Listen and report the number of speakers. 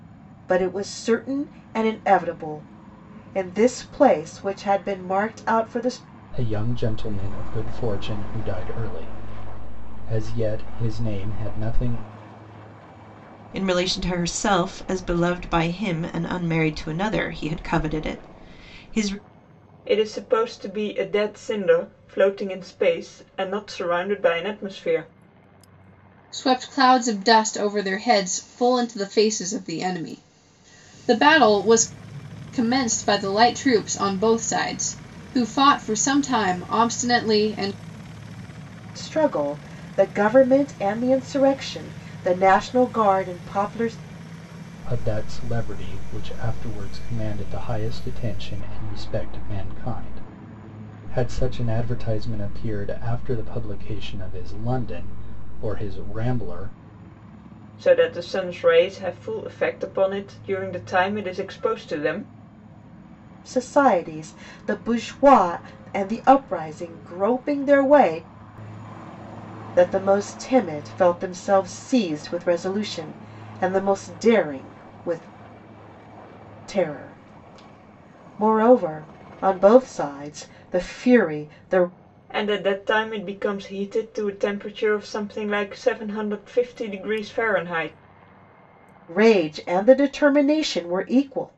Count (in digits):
5